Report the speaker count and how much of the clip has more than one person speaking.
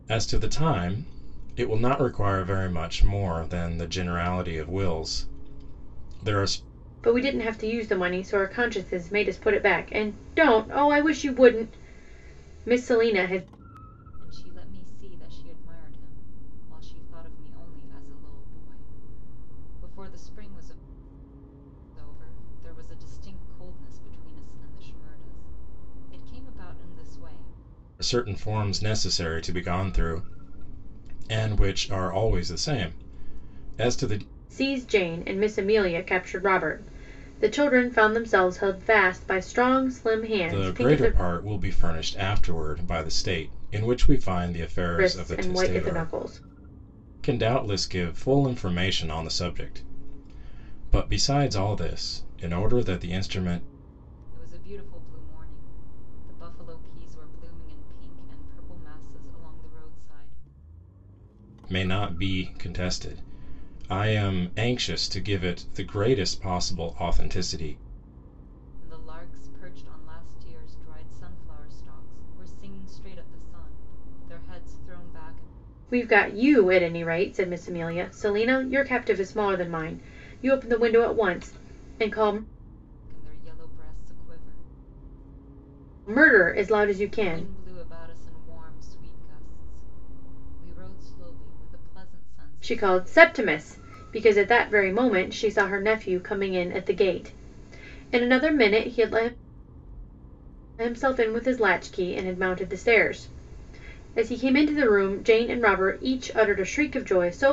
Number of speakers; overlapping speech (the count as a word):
three, about 3%